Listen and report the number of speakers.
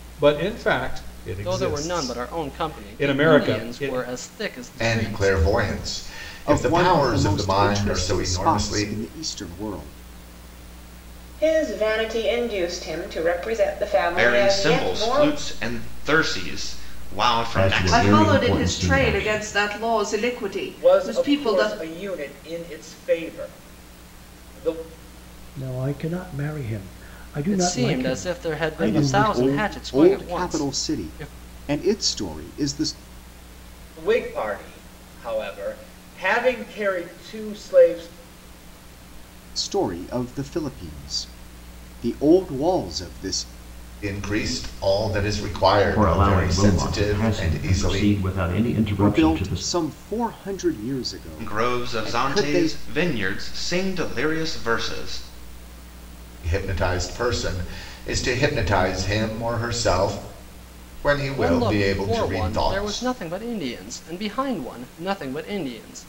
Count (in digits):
10